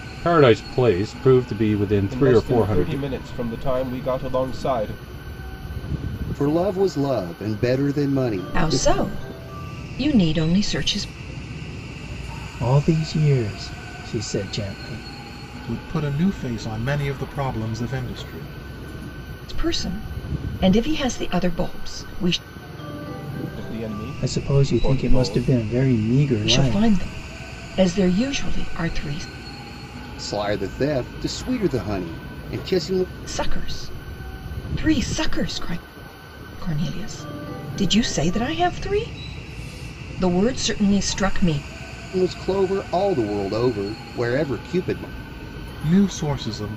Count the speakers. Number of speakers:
6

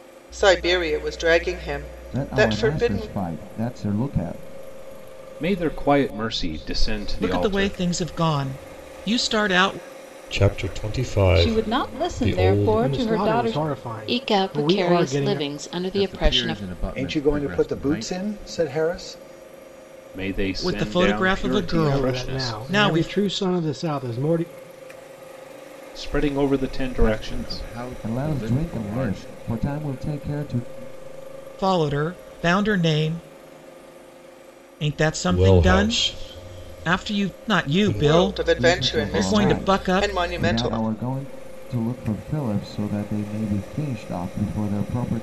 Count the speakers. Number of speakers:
10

